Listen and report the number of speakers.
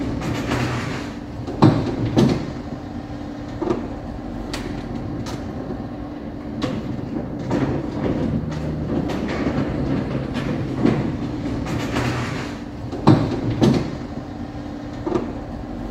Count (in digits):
0